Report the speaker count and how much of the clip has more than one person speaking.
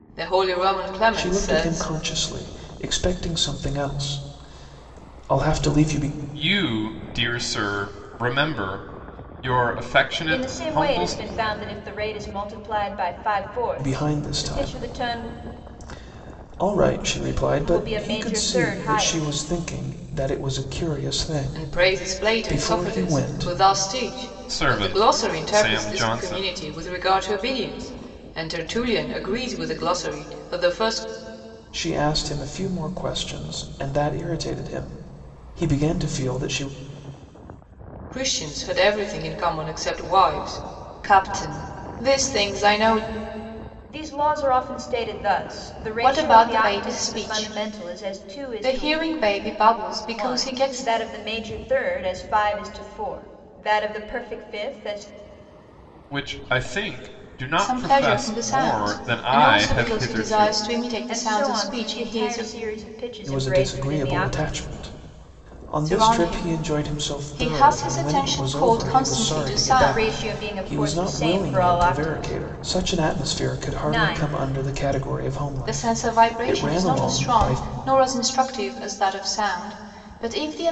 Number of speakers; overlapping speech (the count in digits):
4, about 36%